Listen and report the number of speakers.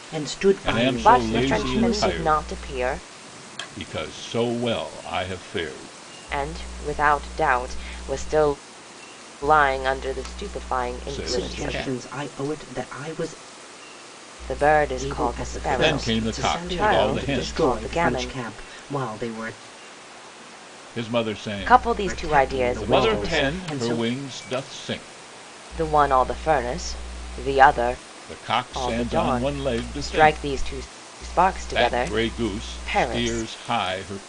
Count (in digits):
3